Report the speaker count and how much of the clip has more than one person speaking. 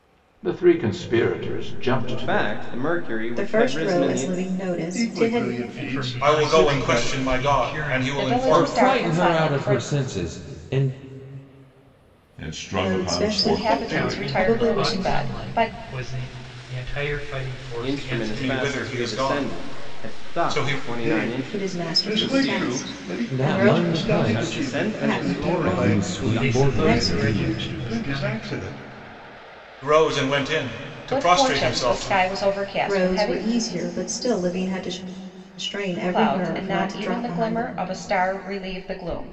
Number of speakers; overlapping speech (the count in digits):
10, about 63%